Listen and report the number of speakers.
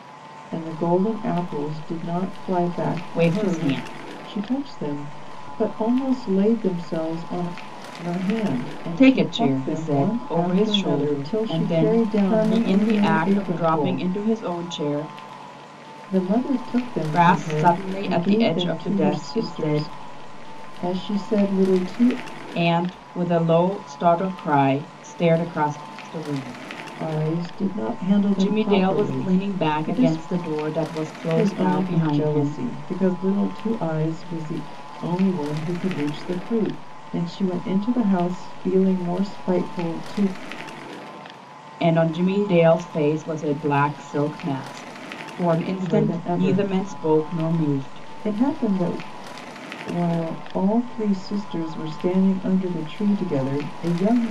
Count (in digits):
2